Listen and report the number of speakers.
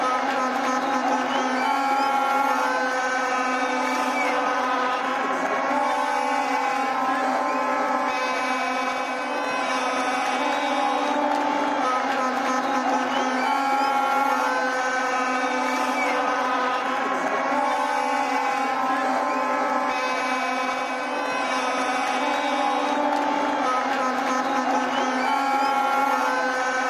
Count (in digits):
0